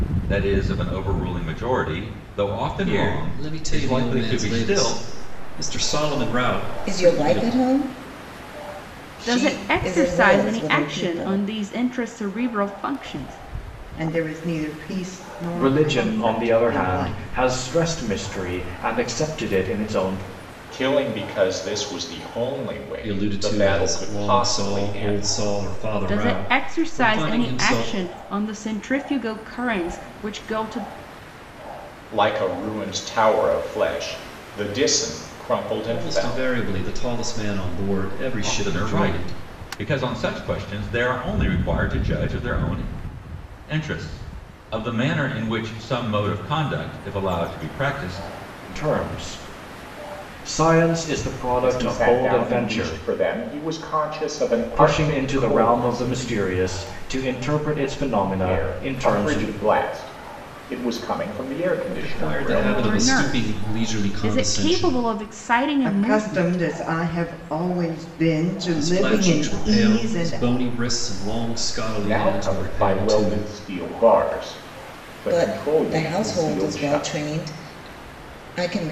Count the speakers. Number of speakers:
7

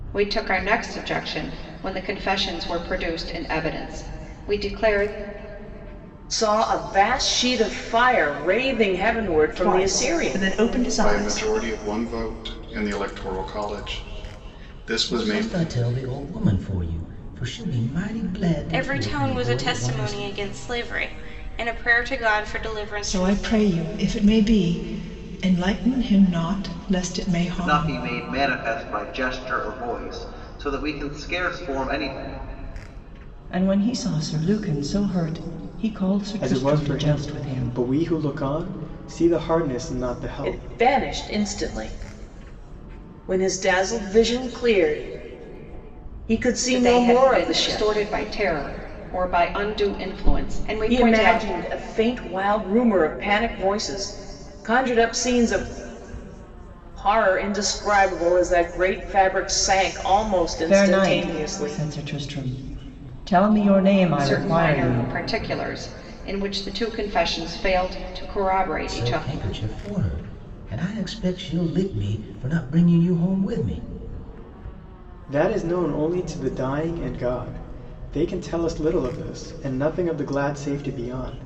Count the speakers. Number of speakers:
10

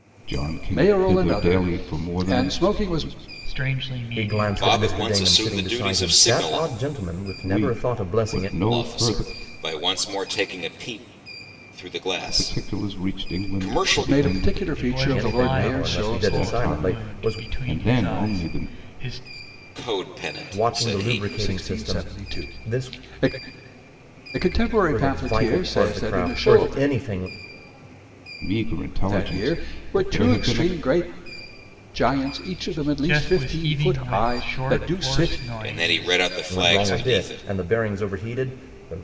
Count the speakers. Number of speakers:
5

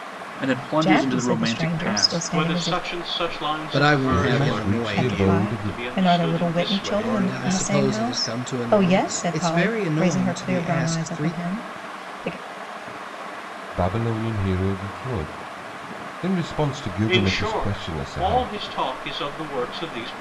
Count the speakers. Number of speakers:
5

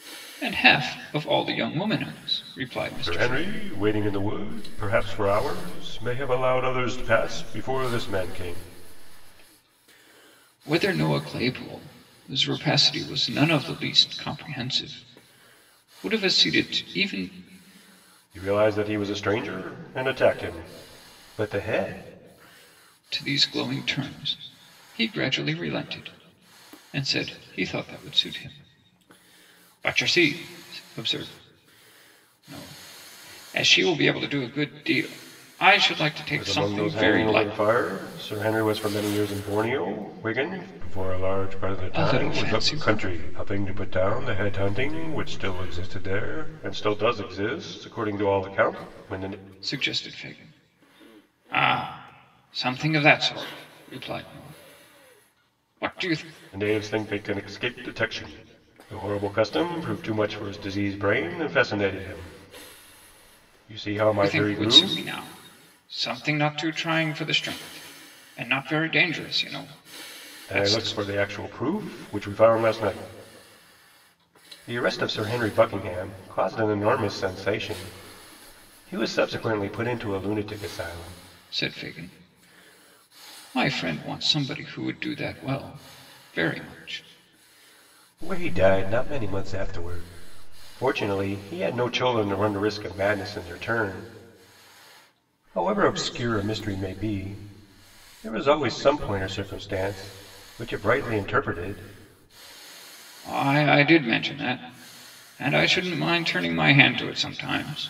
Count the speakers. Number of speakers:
2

